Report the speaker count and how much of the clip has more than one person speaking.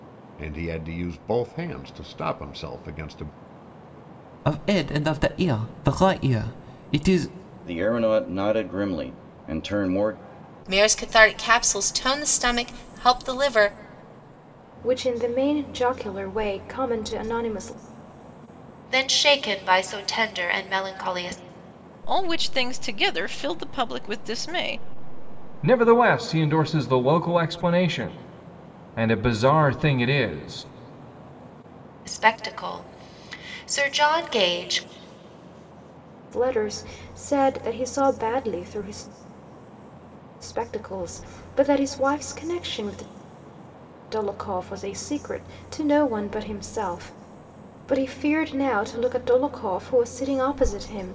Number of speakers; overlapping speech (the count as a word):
eight, no overlap